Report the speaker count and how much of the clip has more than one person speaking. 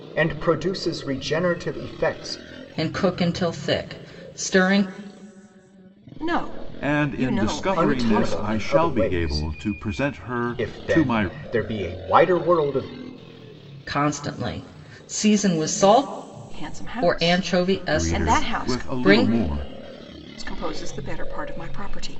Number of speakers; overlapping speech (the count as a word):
four, about 26%